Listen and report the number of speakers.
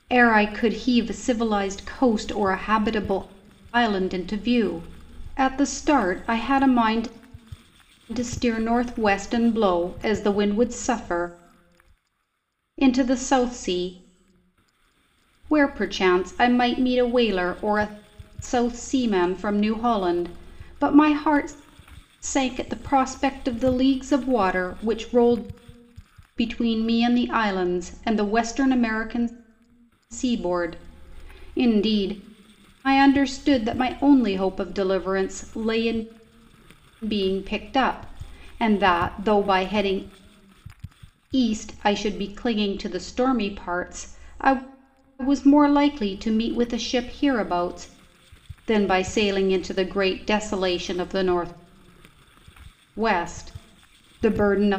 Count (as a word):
one